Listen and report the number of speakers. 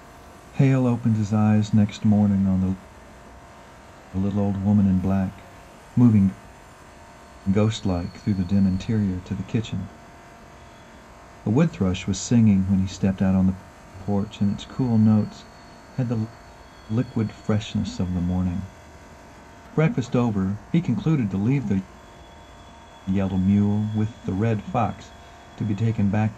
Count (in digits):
1